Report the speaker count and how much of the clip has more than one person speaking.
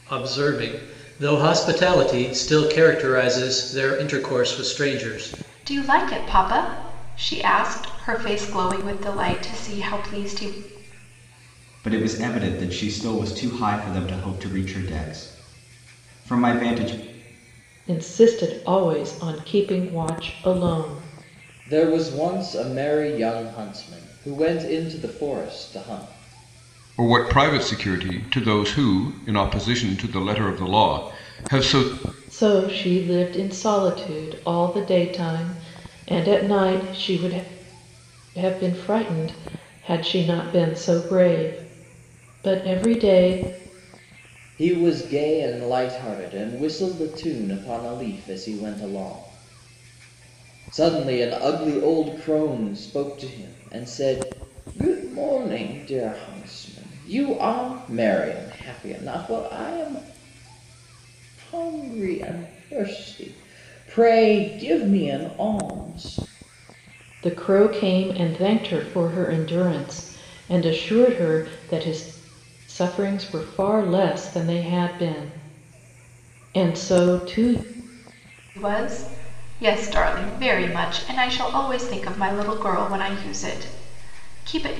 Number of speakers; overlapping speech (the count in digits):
6, no overlap